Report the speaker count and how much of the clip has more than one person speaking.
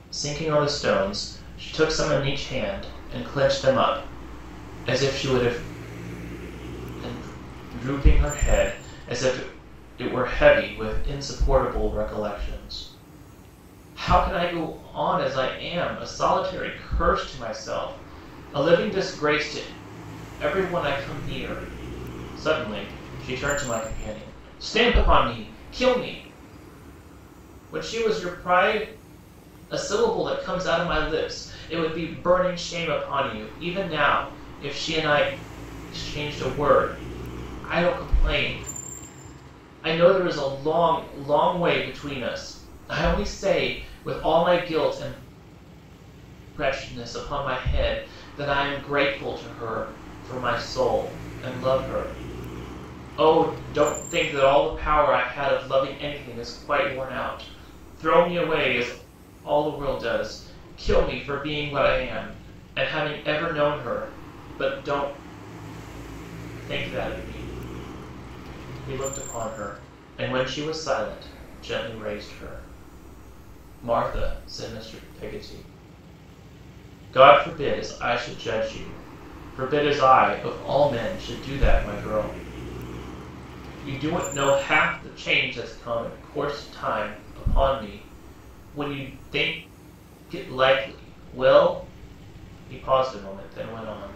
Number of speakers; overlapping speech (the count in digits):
1, no overlap